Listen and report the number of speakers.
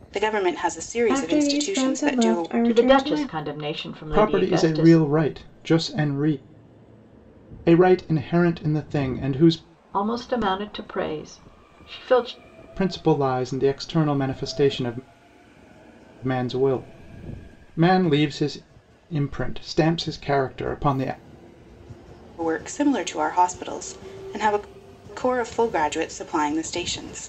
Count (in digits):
4